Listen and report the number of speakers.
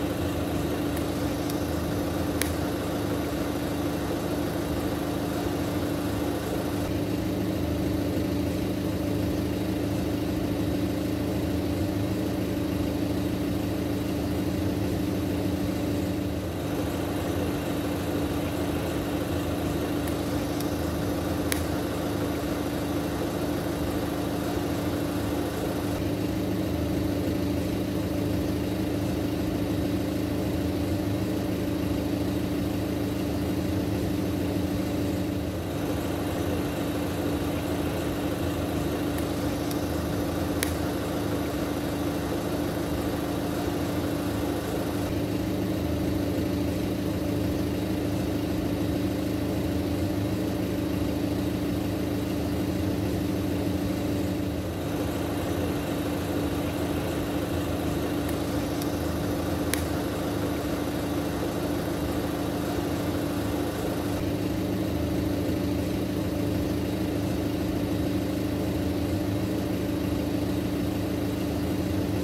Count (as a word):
zero